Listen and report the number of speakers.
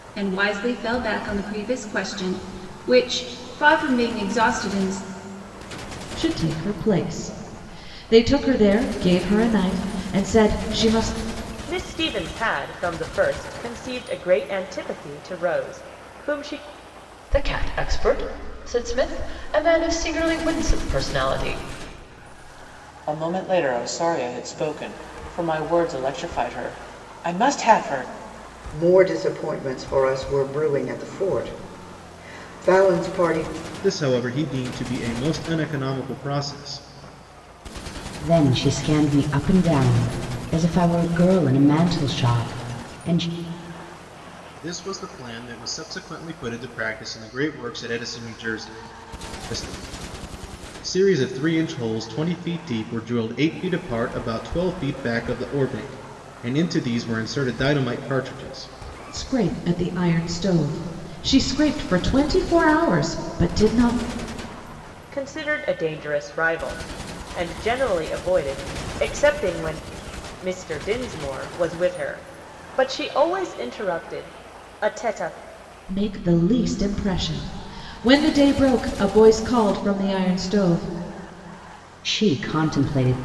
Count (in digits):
8